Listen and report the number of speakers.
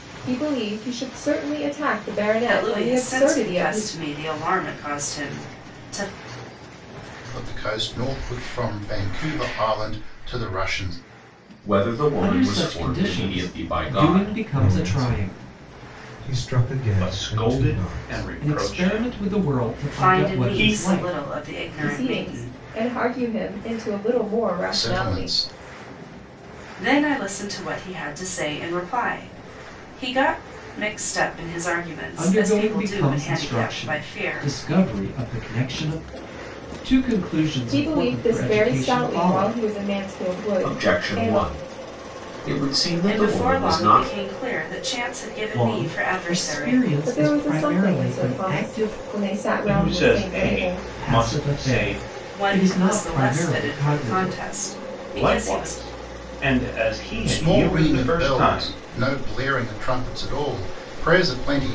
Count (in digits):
7